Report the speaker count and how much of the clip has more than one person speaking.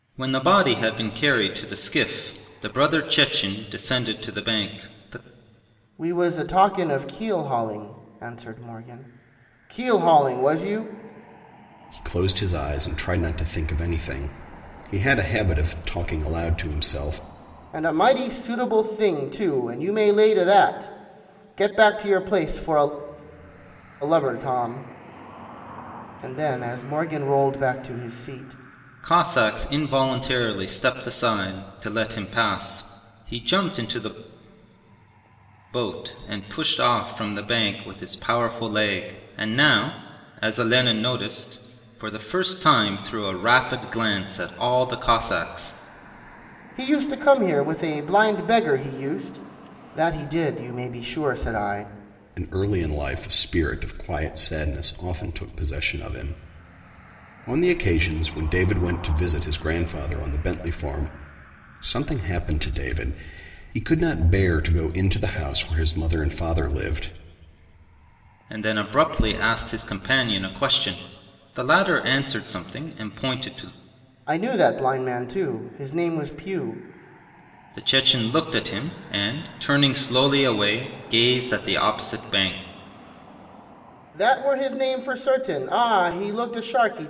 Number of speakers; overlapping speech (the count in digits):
3, no overlap